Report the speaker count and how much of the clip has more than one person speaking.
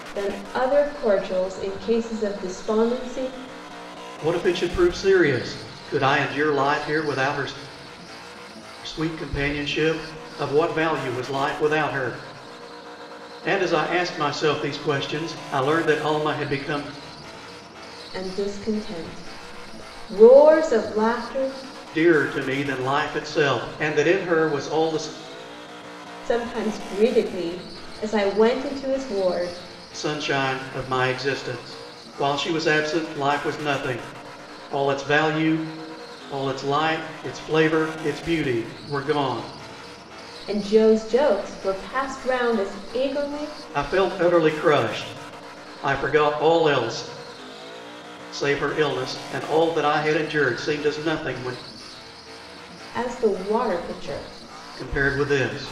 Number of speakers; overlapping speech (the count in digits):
2, no overlap